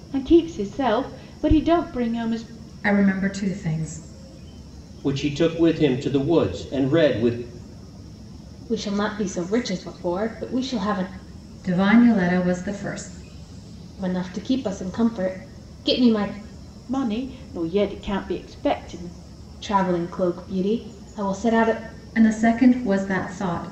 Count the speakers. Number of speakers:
4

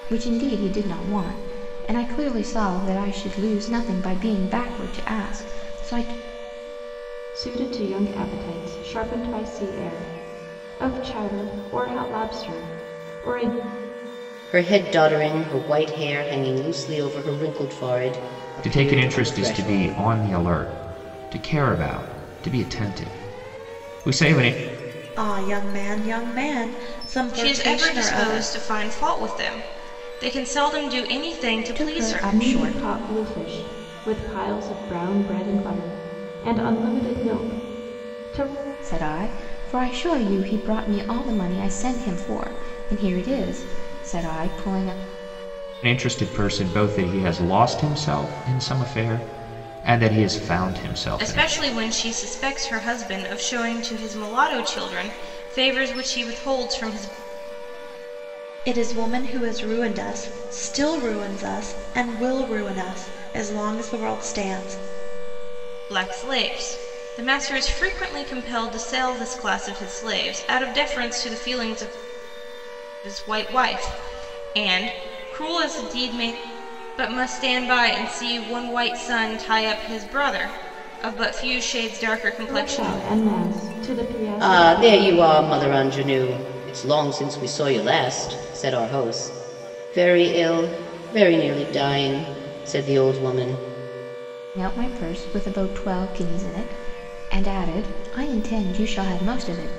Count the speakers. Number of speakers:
6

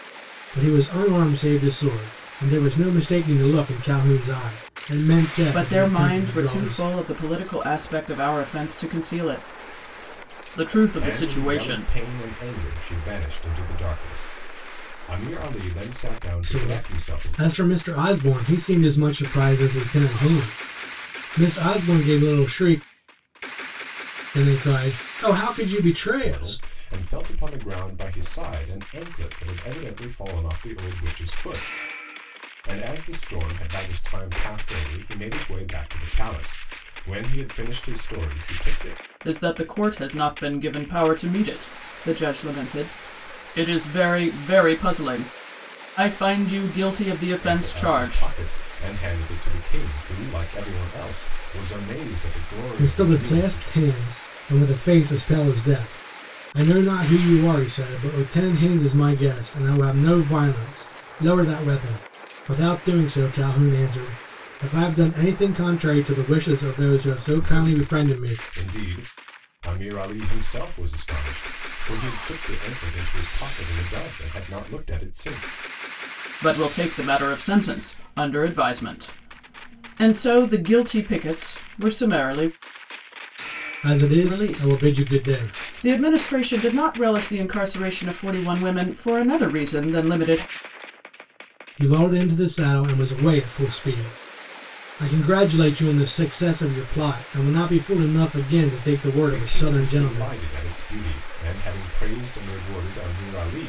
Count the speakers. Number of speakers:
3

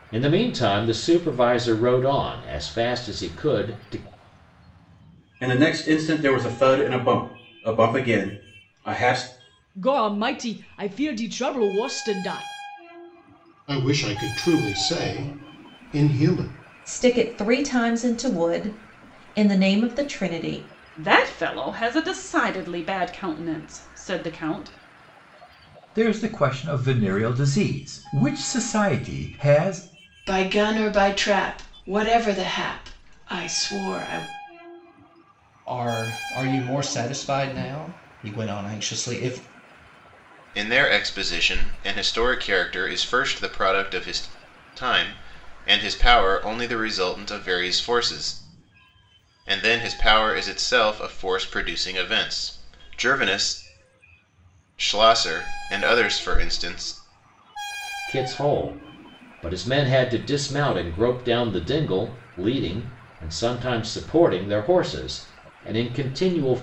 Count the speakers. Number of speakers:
10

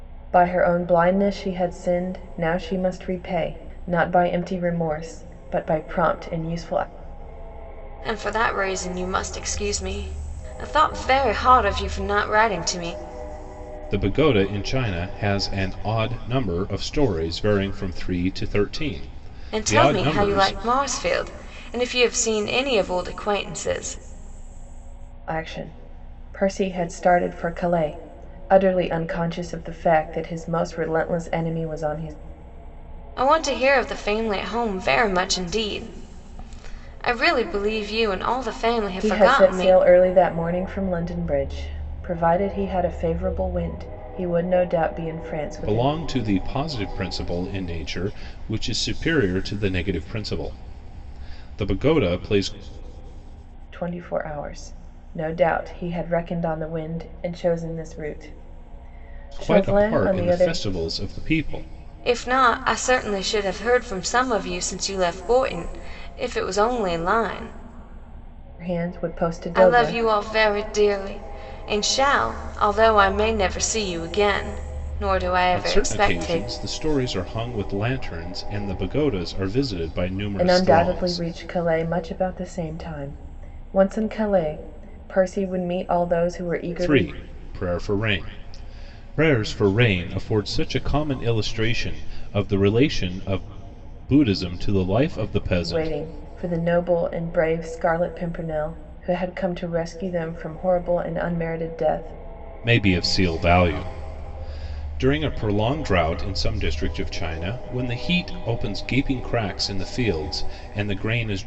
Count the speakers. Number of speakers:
3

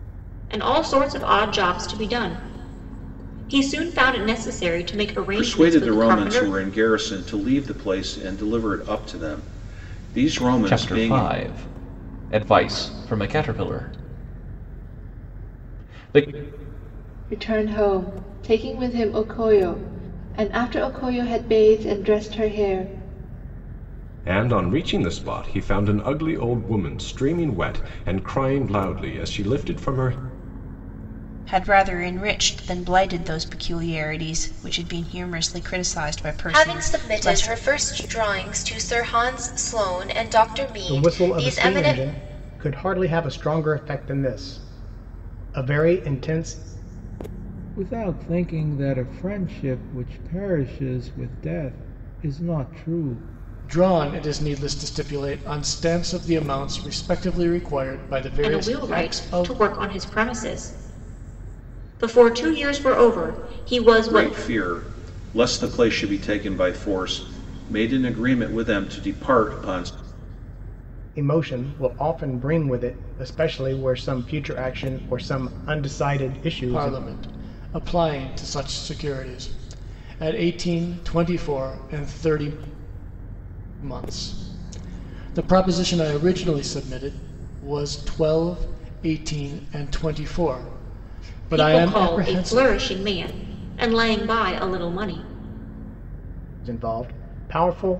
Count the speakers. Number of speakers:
10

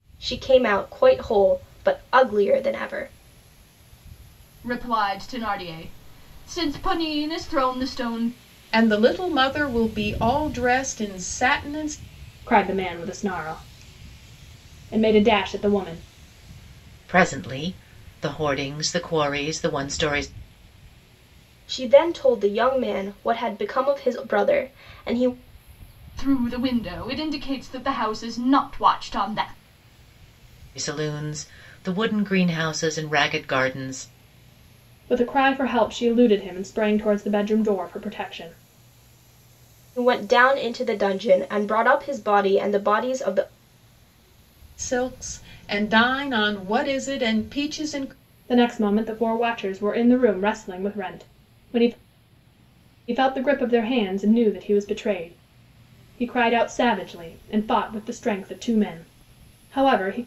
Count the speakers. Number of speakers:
5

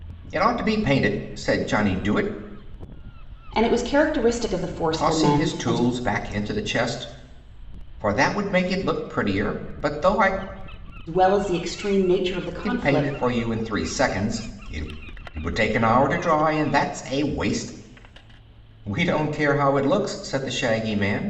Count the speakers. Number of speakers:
2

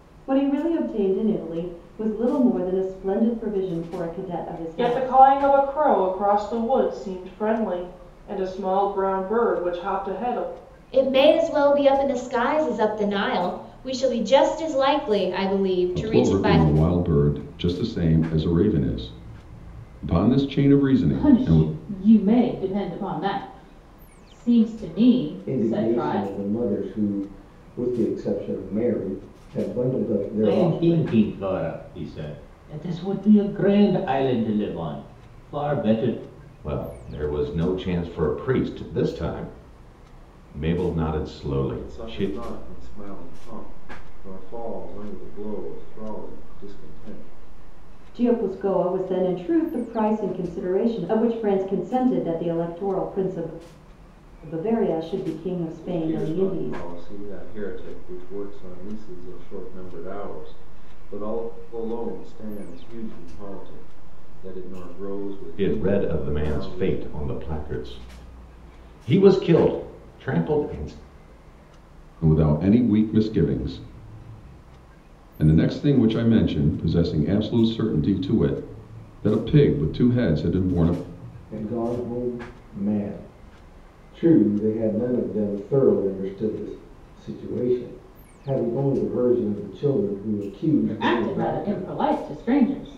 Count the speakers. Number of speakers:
9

